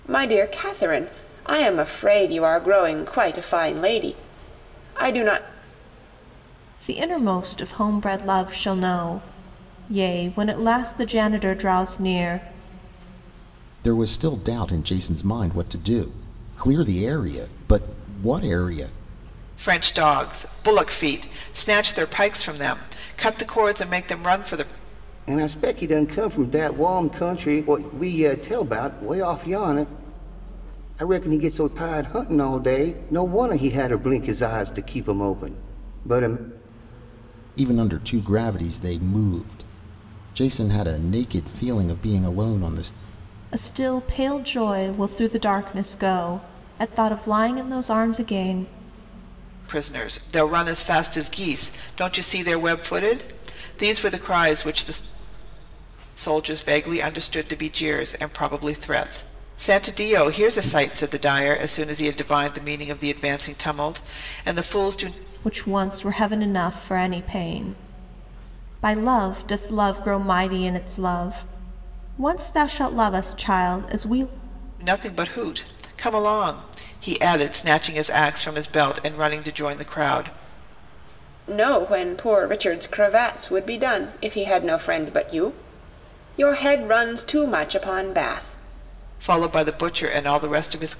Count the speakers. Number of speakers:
5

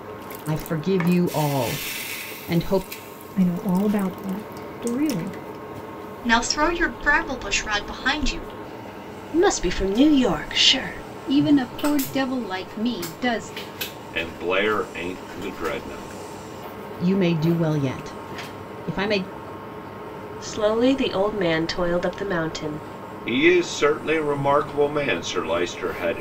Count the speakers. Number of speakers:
6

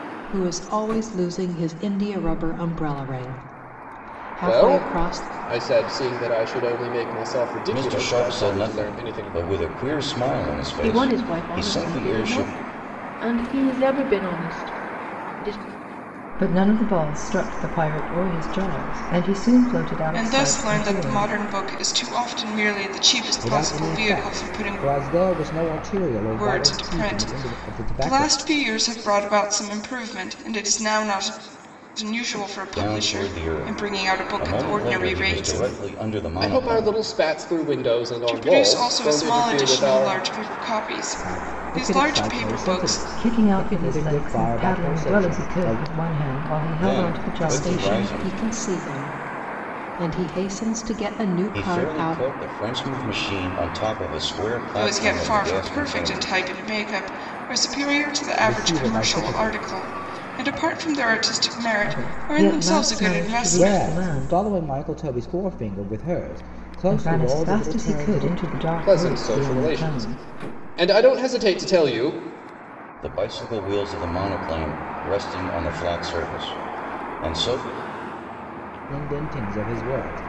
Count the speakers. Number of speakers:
7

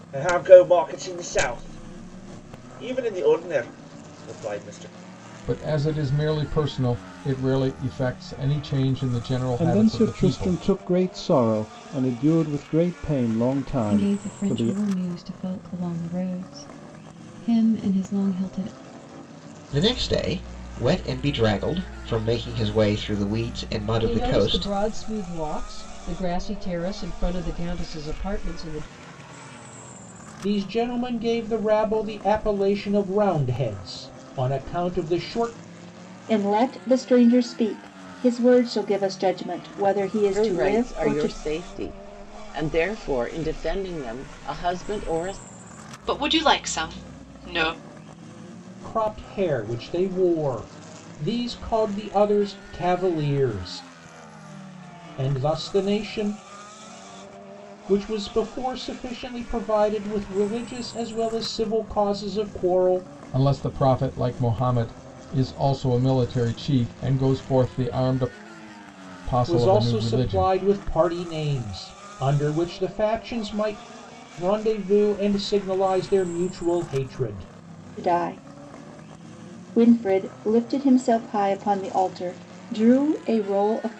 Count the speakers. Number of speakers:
10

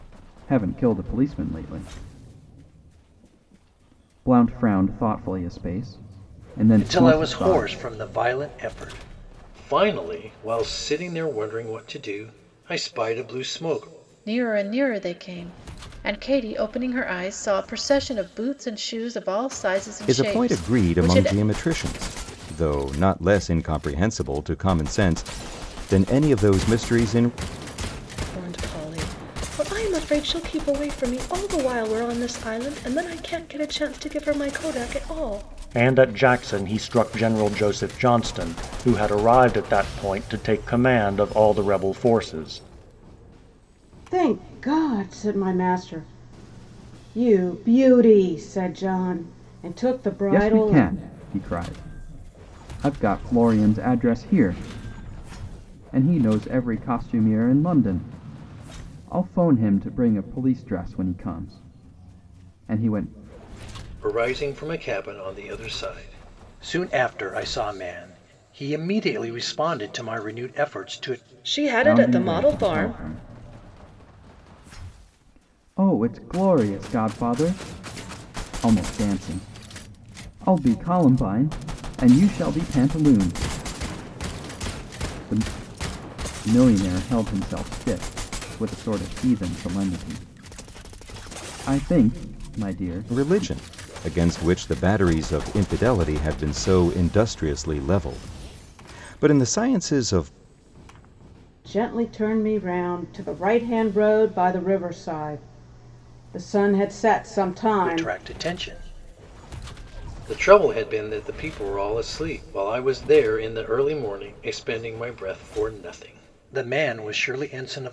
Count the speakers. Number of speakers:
7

